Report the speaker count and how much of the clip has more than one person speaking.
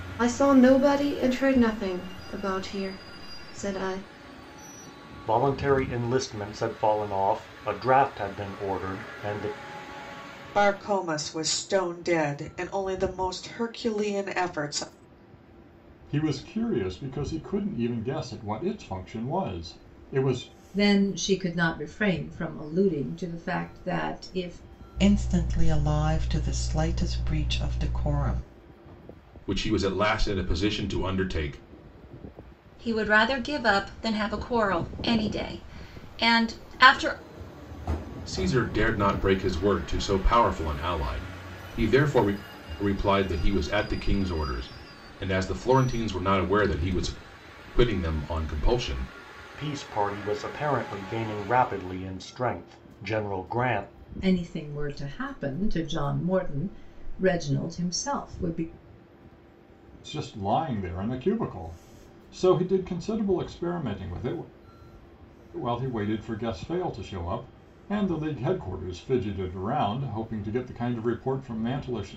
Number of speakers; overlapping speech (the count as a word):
eight, no overlap